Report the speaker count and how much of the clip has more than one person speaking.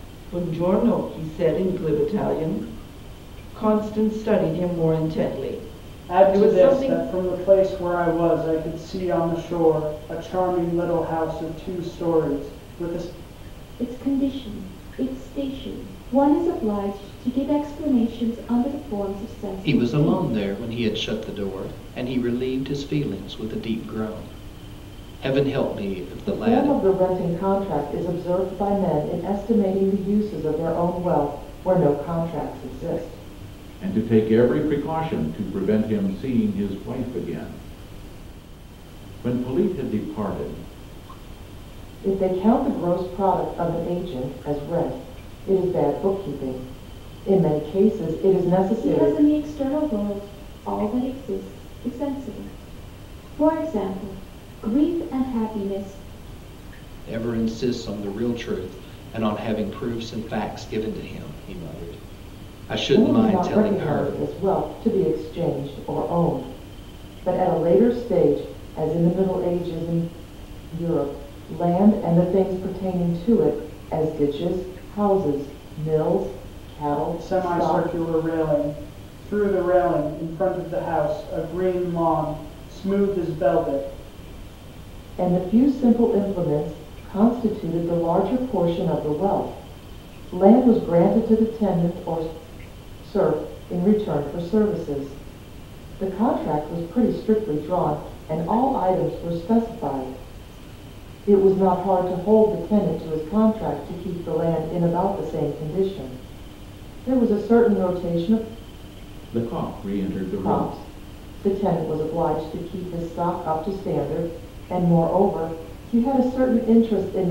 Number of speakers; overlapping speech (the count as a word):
six, about 5%